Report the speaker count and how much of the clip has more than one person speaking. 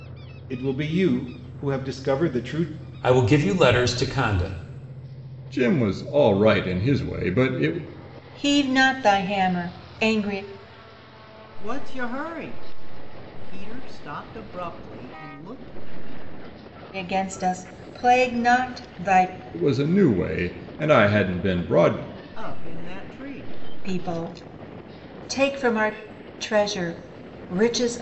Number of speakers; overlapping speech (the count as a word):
five, no overlap